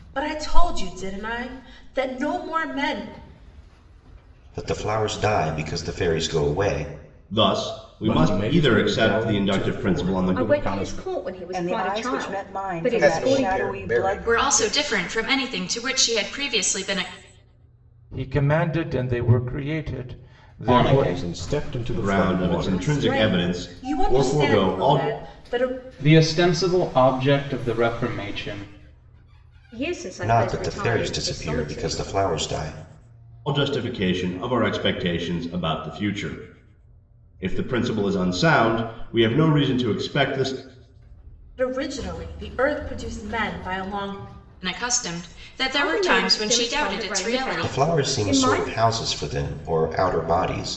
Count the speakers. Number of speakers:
10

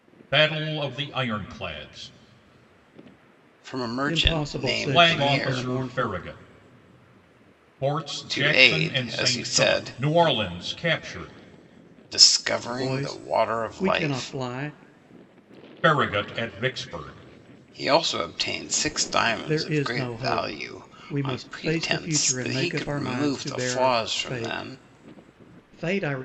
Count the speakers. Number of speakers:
3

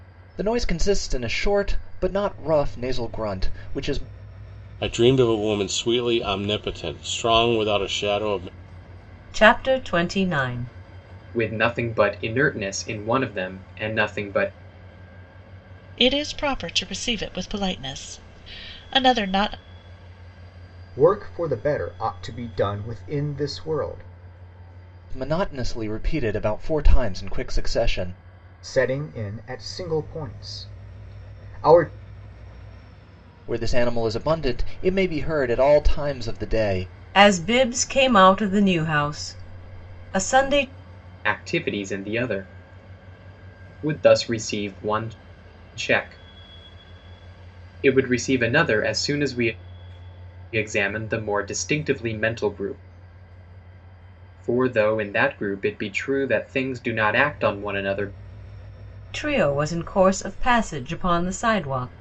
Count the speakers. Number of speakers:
6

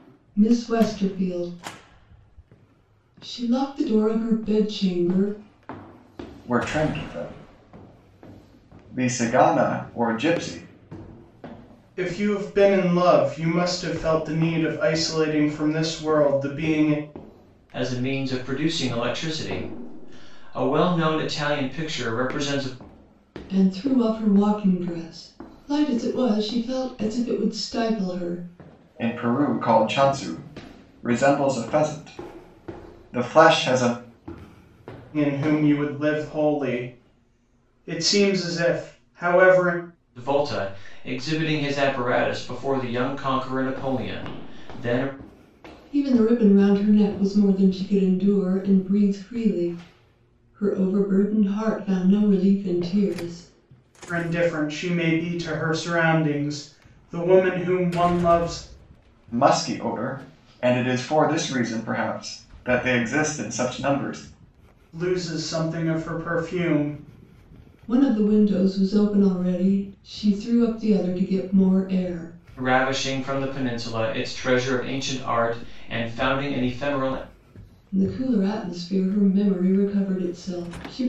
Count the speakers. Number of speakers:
4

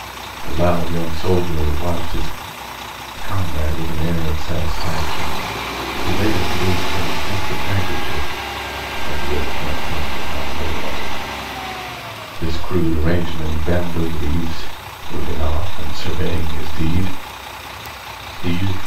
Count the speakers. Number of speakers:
1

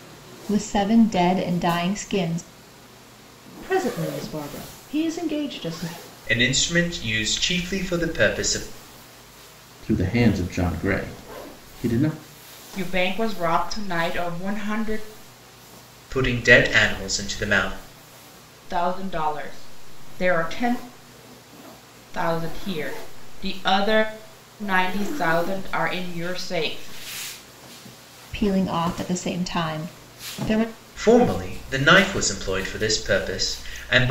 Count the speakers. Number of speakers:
5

